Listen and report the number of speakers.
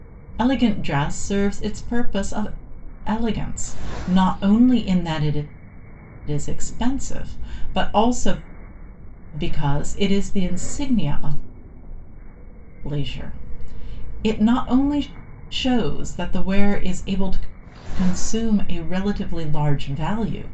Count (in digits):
1